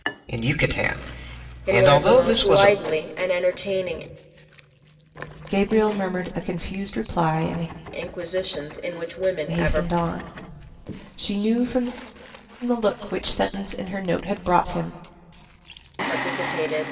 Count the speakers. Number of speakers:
3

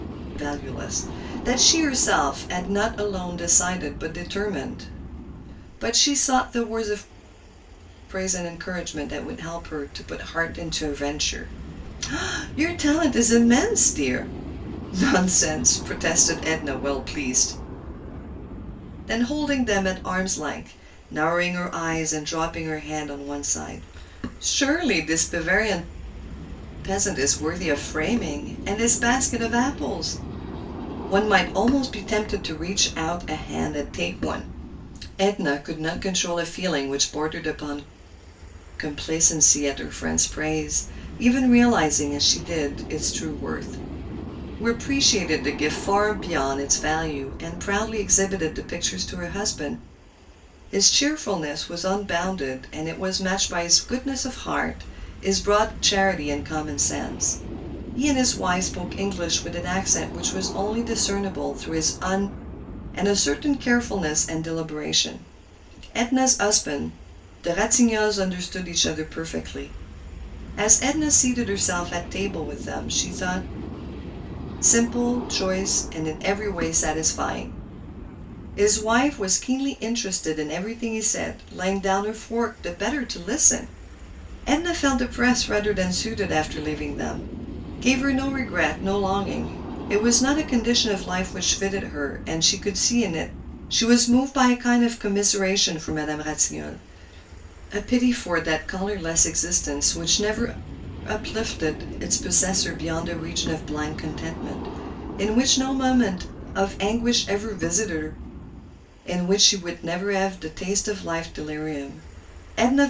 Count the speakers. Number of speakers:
1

